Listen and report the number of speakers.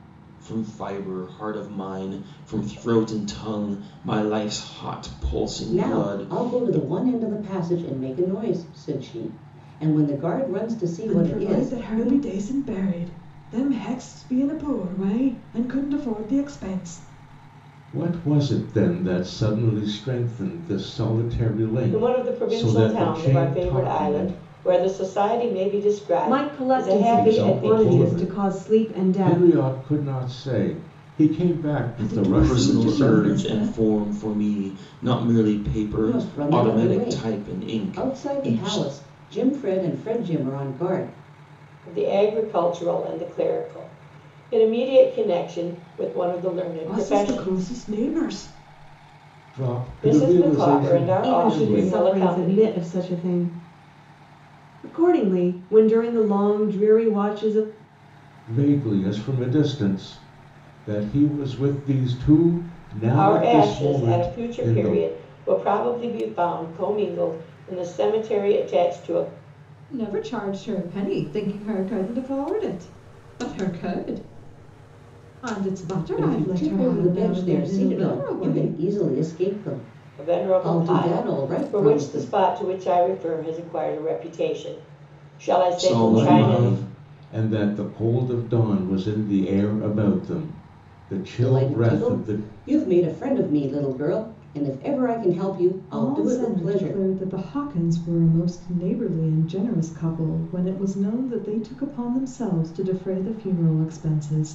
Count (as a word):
six